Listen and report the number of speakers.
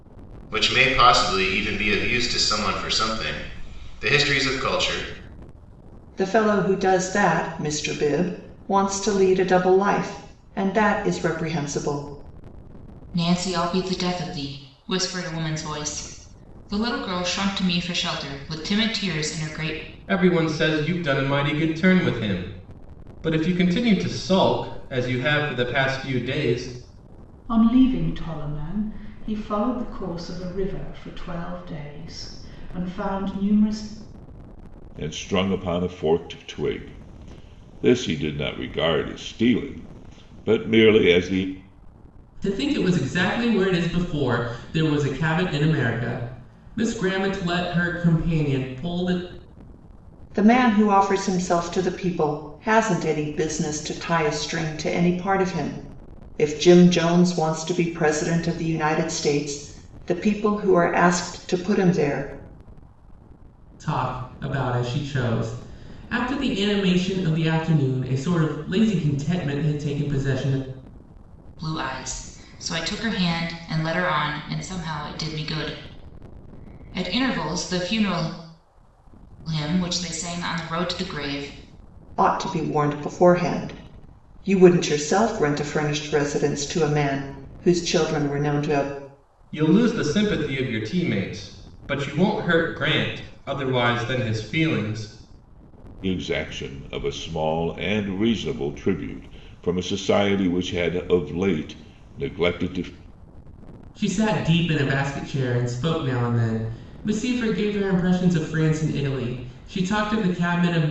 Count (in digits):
7